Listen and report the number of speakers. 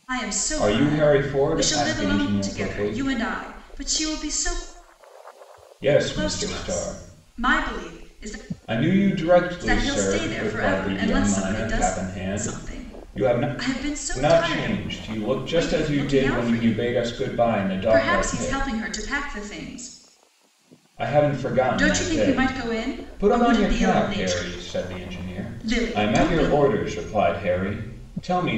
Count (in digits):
2